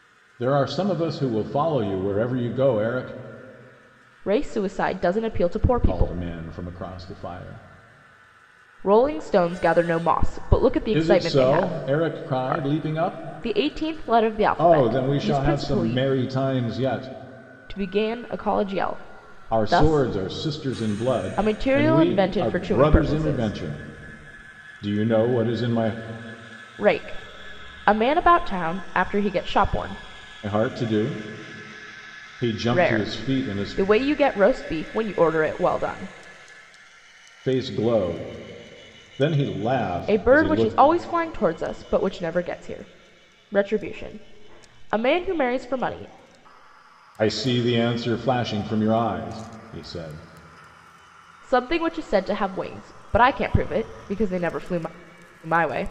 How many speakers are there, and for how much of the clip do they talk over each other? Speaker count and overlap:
2, about 15%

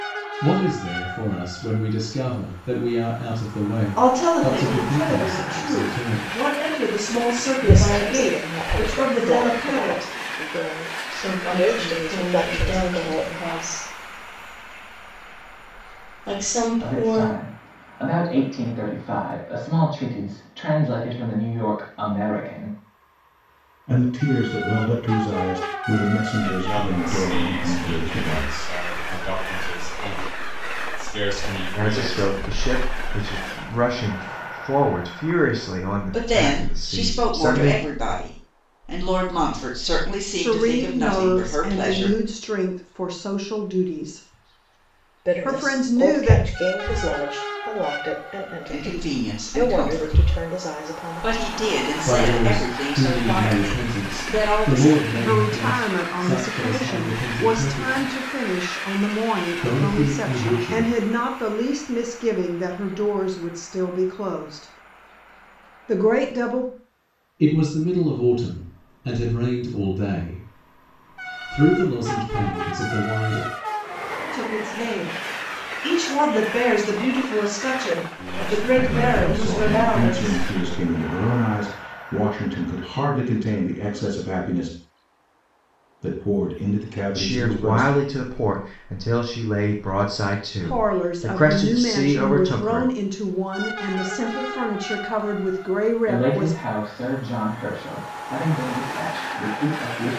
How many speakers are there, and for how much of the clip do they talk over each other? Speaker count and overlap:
10, about 32%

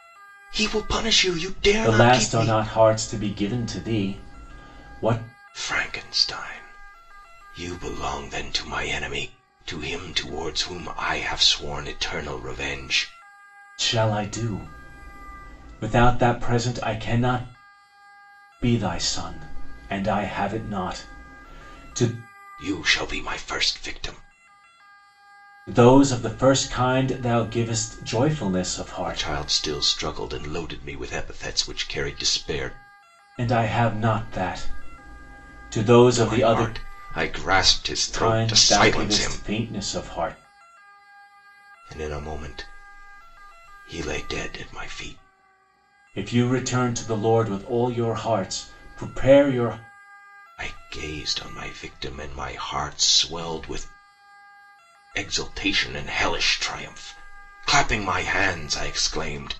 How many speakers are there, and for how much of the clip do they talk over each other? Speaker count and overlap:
2, about 5%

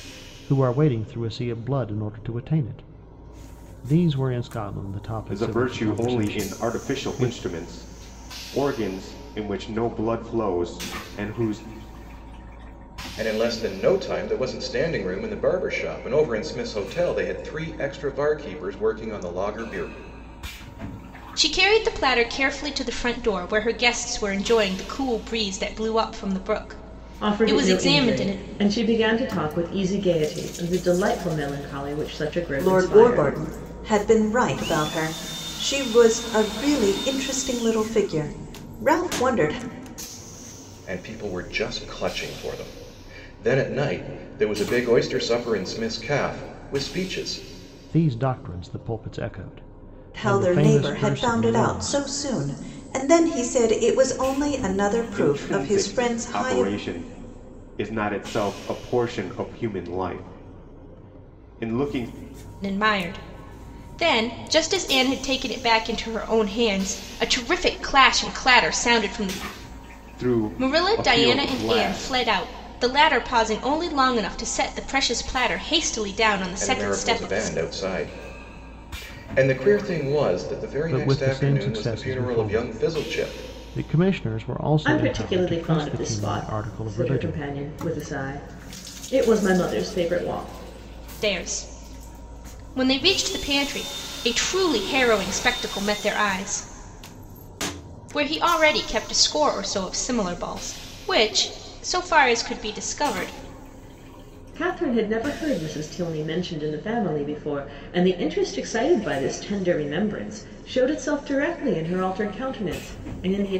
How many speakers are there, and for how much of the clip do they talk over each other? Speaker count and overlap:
6, about 14%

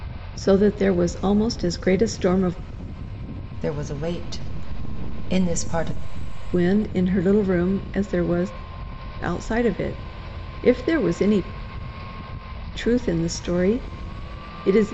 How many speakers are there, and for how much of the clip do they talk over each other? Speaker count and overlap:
2, no overlap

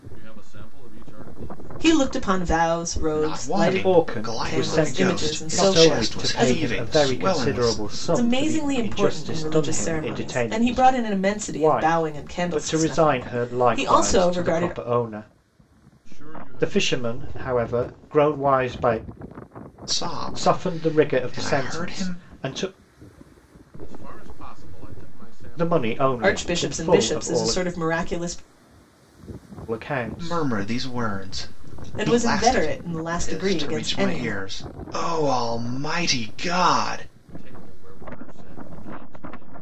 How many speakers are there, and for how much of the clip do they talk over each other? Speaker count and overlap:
4, about 51%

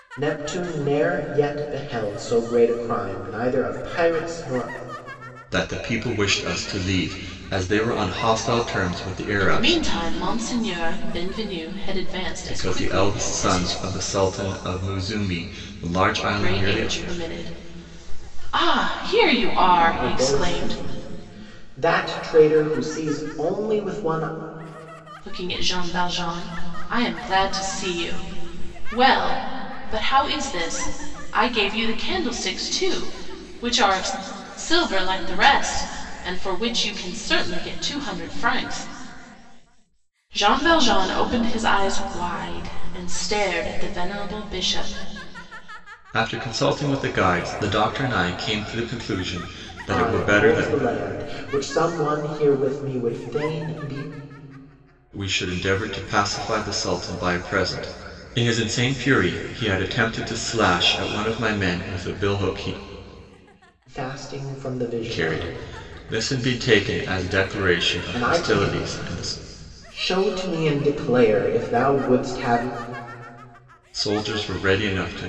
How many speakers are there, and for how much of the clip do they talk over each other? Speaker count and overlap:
3, about 8%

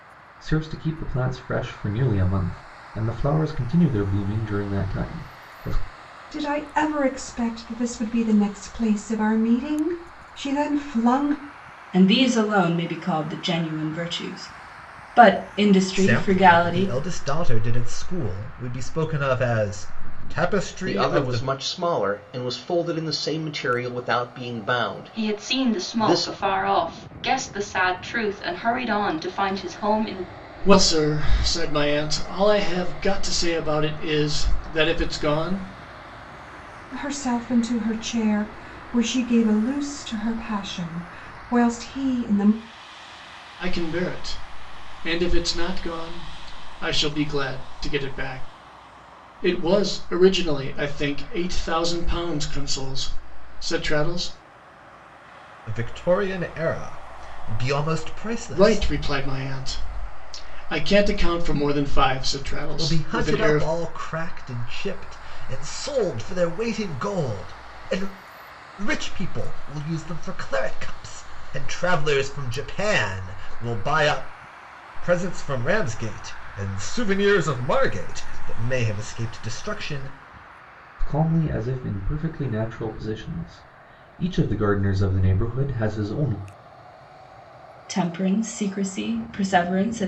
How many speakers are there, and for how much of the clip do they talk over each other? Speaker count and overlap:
7, about 5%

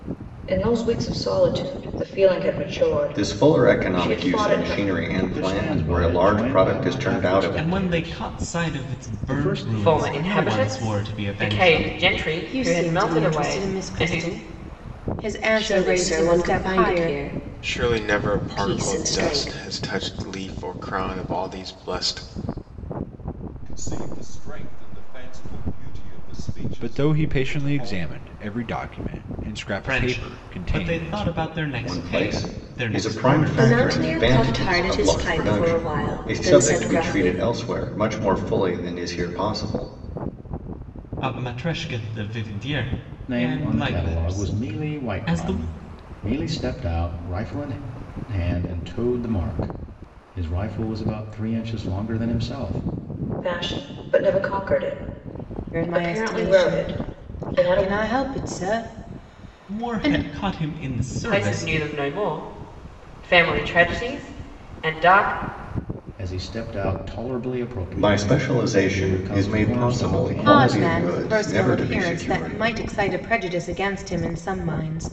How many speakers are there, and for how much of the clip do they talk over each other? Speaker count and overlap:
10, about 44%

